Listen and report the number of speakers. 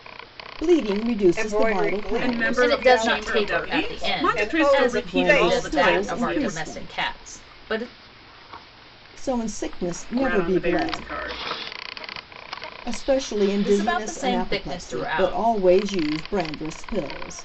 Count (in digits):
4